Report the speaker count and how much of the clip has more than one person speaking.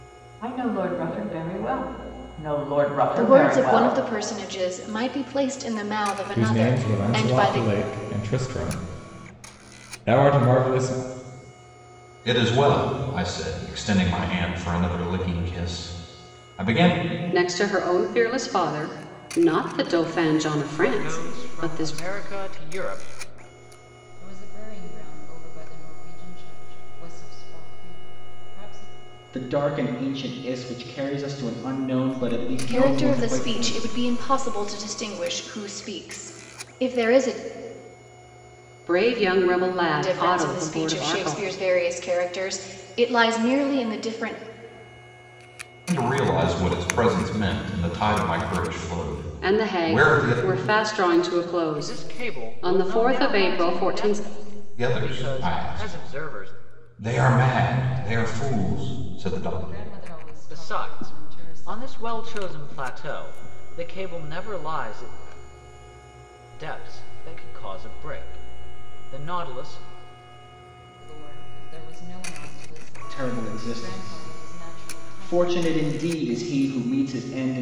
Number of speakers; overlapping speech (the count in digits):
8, about 25%